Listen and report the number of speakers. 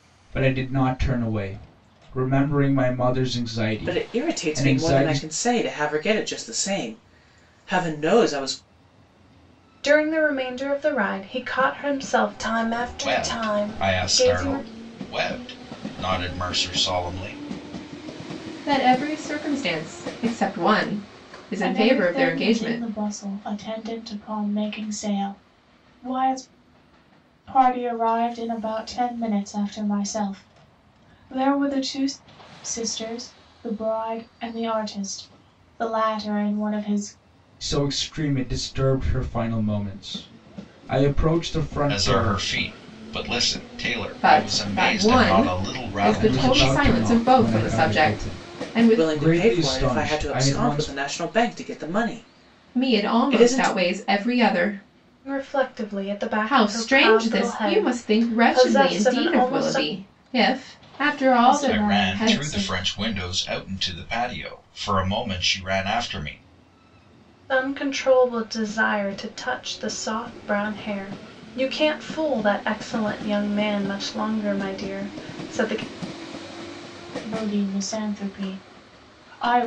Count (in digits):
6